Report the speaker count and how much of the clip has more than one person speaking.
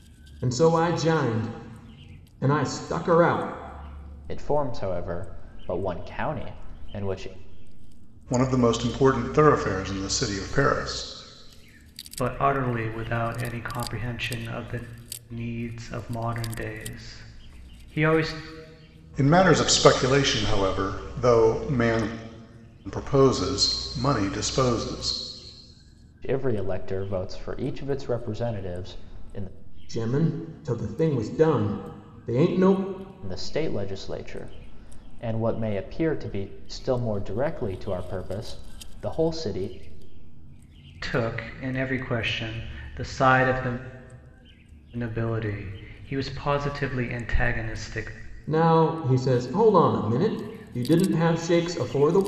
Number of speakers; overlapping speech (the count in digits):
4, no overlap